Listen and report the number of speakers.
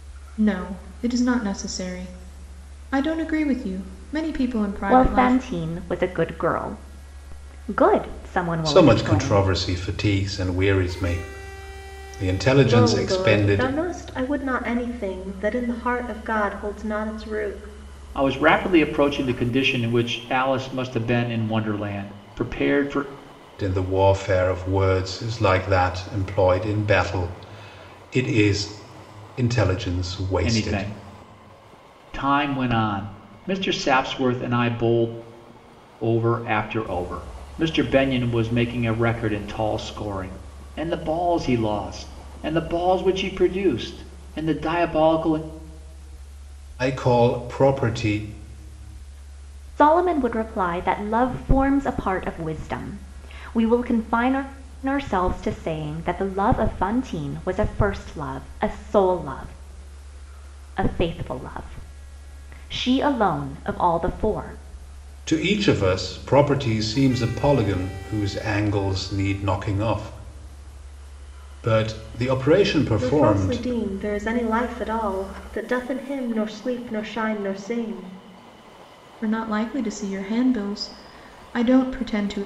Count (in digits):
5